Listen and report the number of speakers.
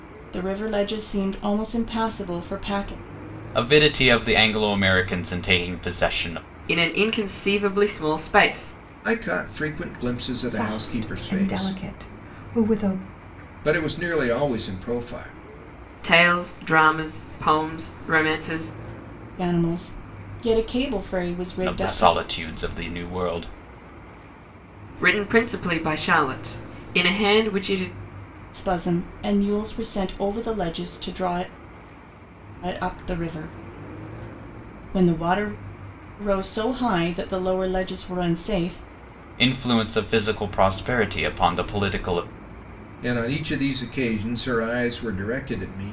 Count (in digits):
5